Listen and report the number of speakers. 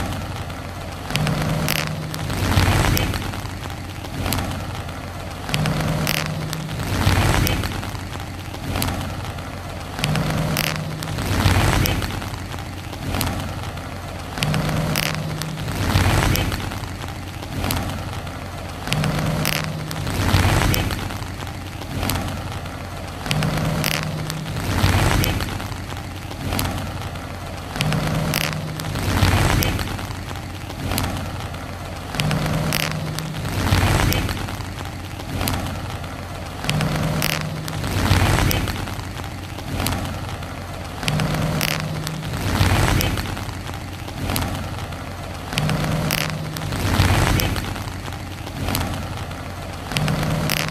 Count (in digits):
0